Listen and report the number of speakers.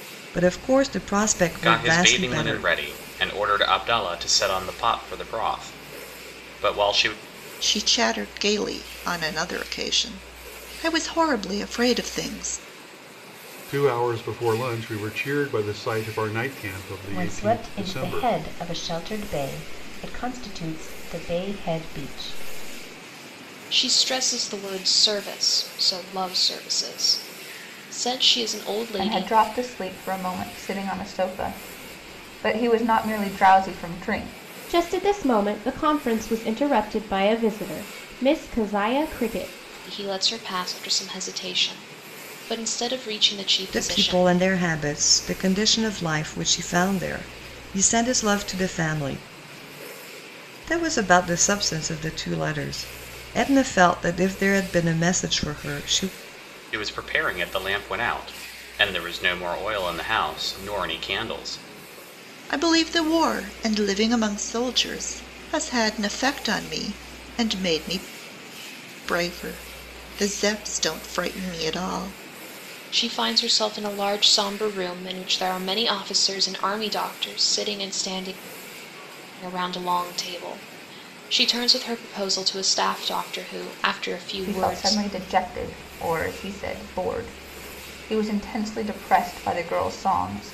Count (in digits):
8